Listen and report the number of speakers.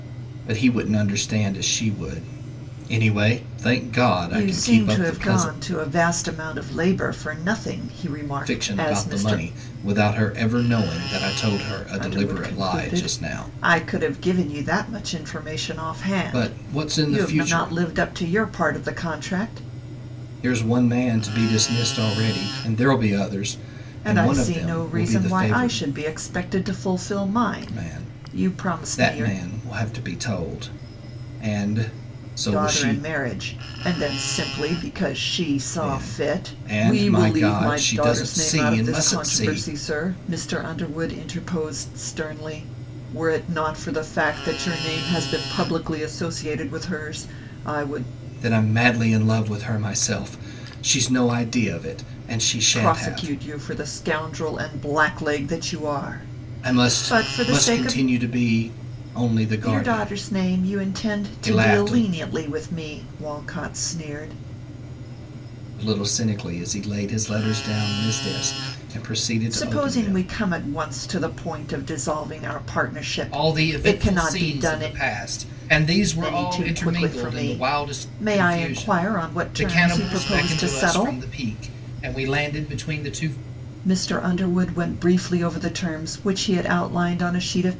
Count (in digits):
2